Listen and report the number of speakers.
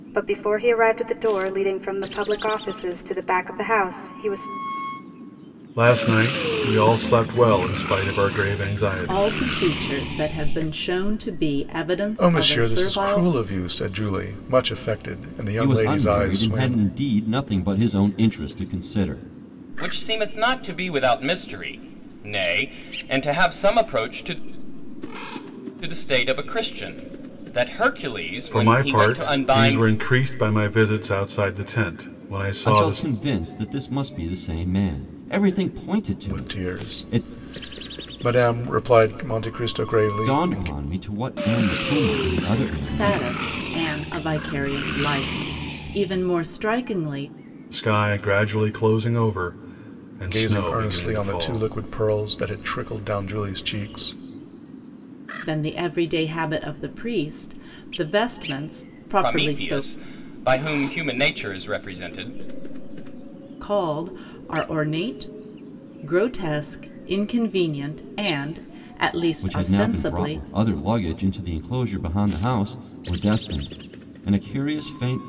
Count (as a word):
six